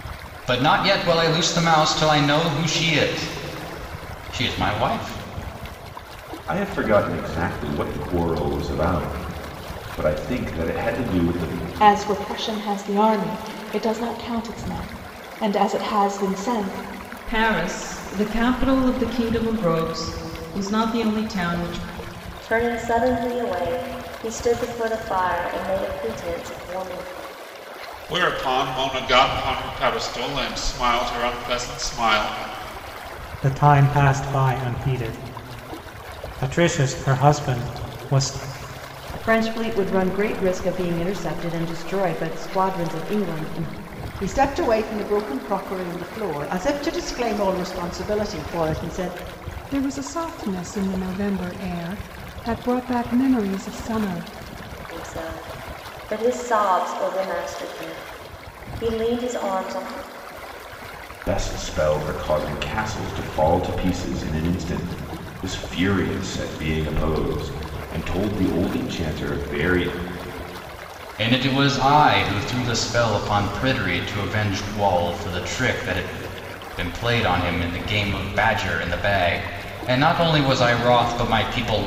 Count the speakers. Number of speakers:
10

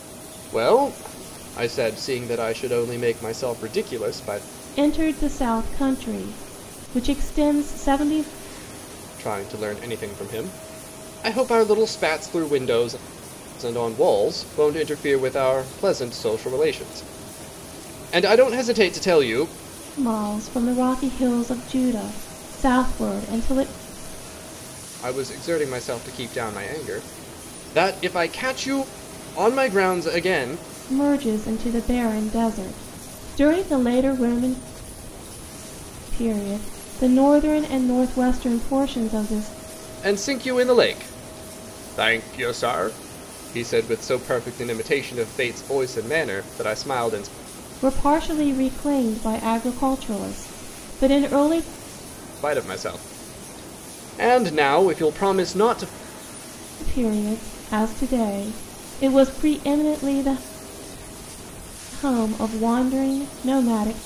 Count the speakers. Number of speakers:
2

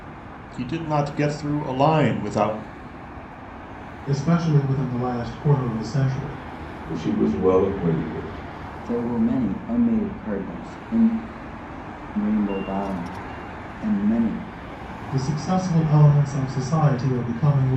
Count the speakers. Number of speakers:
4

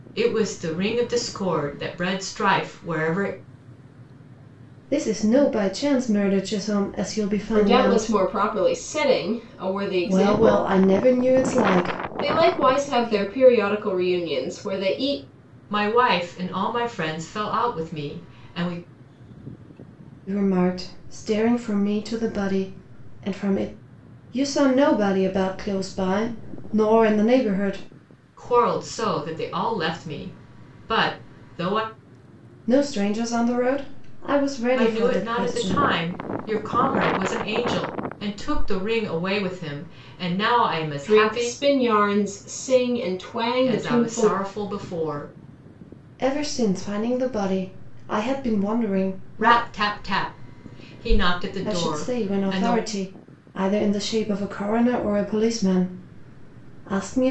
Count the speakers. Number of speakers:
3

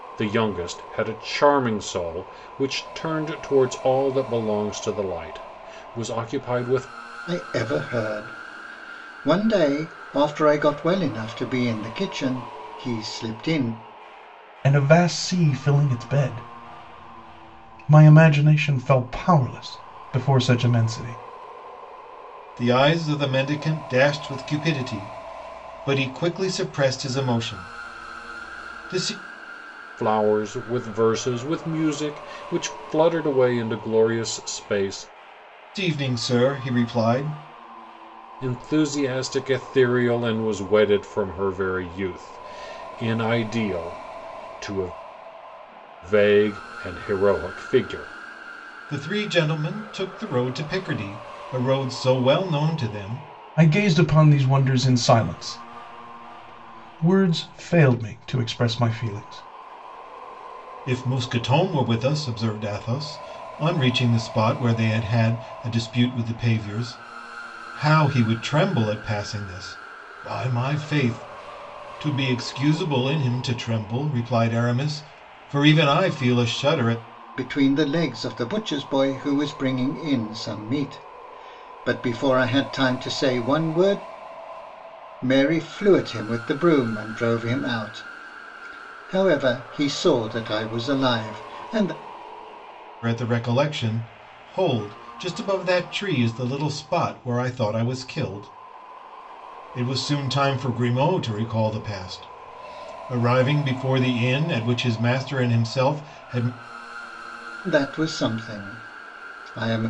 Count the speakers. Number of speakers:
4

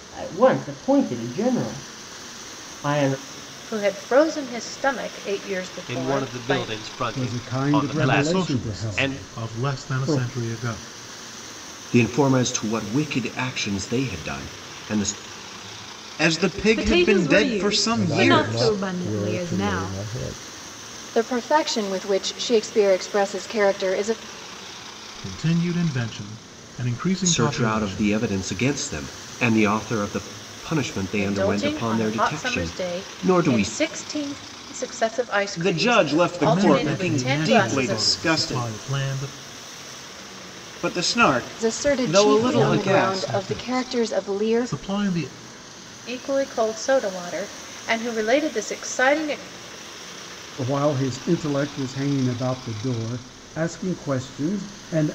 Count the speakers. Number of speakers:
10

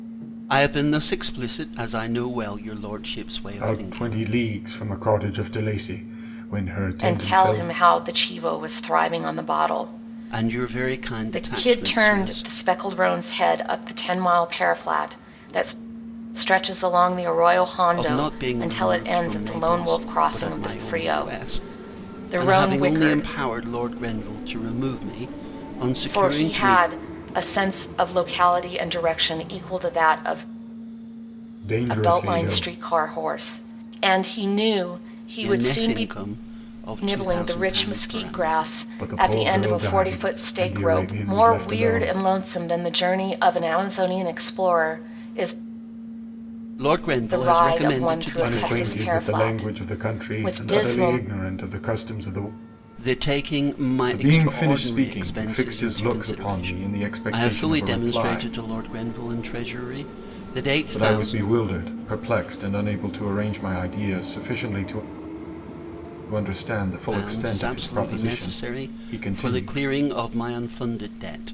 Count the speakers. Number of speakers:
3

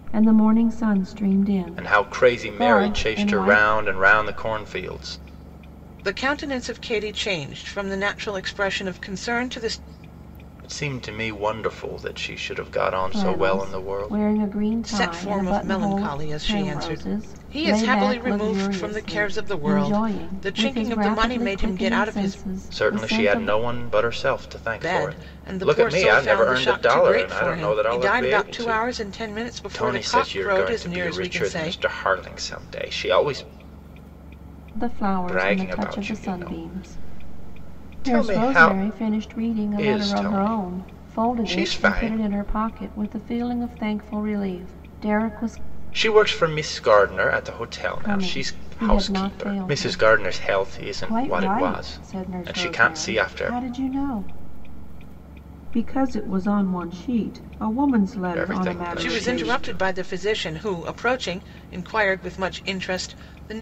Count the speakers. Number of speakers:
3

